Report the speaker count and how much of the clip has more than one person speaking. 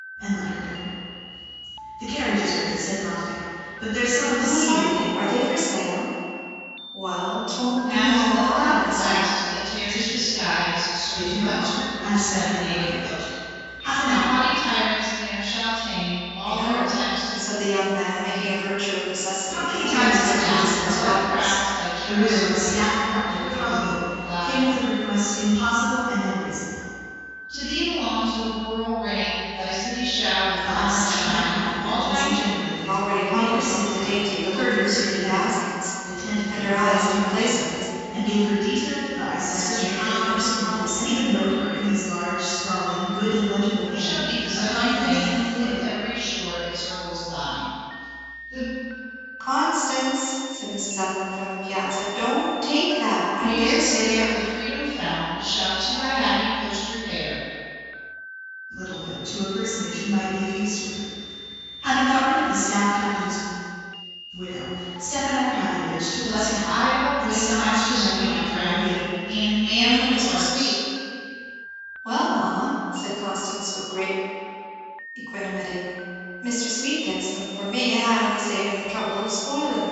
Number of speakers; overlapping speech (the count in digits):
3, about 34%